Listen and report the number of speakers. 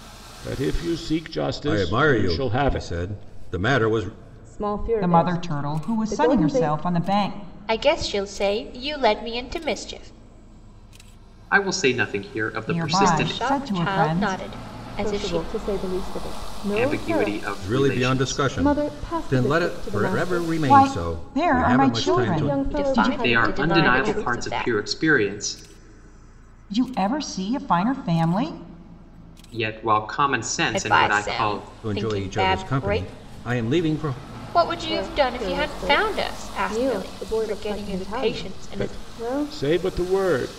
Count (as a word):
six